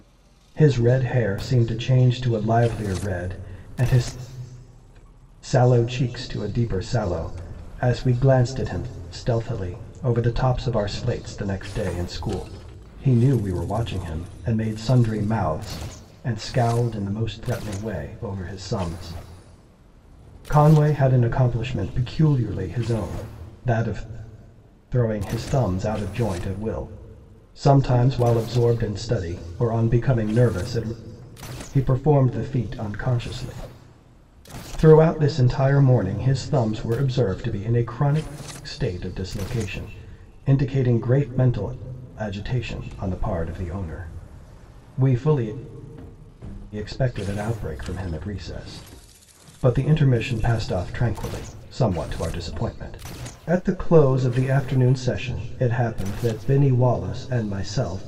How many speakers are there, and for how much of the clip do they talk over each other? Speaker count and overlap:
one, no overlap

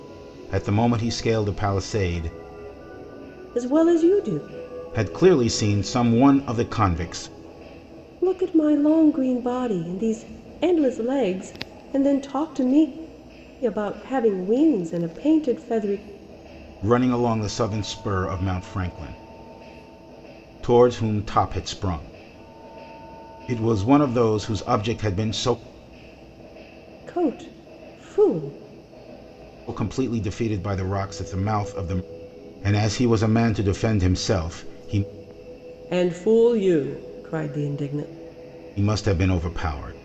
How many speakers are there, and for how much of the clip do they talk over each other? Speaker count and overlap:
two, no overlap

